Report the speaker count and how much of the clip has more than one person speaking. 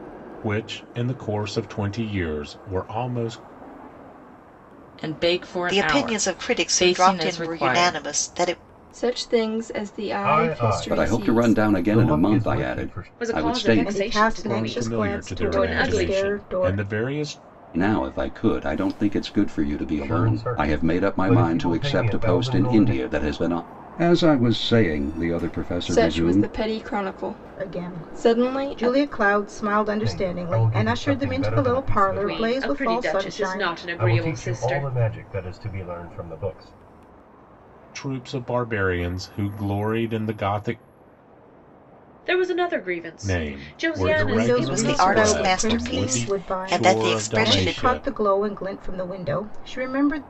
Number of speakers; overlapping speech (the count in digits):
8, about 47%